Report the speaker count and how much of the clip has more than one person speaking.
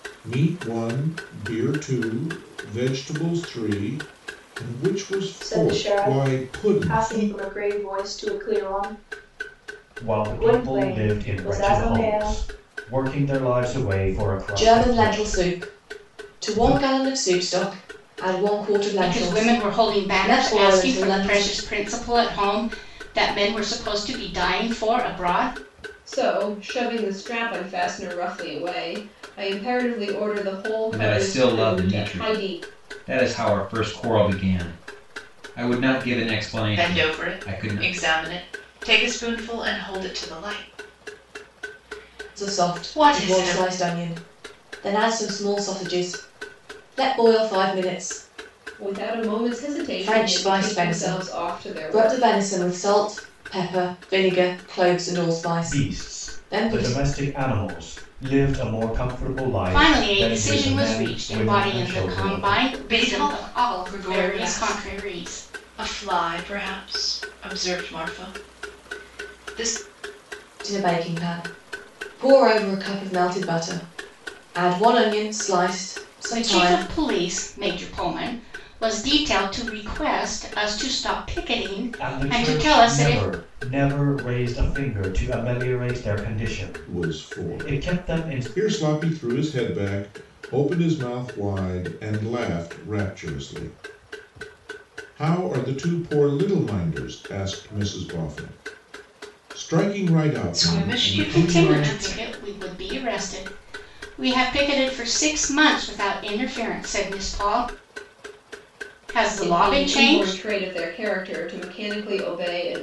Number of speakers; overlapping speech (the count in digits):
8, about 26%